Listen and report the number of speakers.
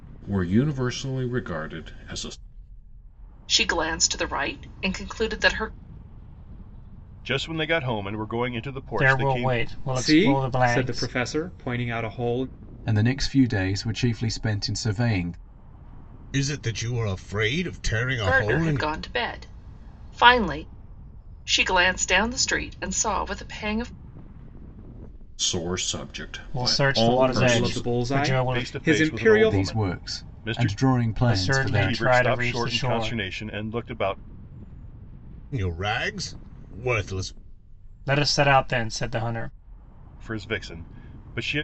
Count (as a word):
seven